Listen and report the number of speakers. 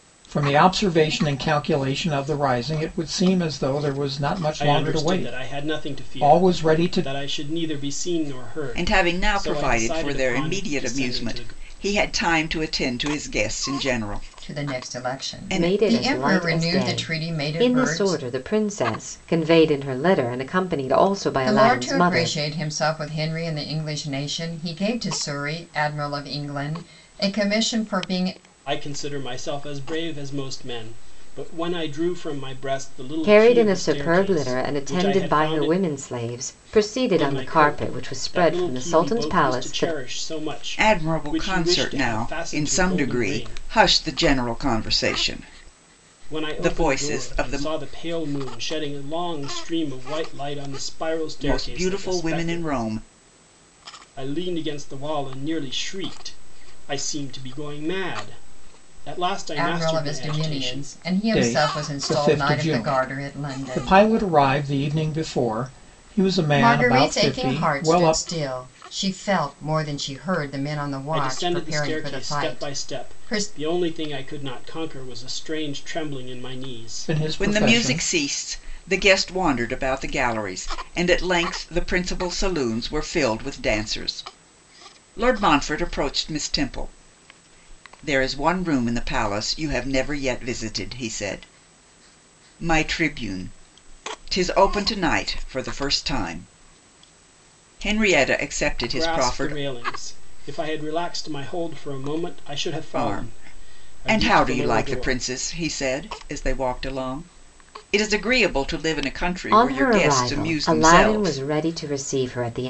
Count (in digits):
5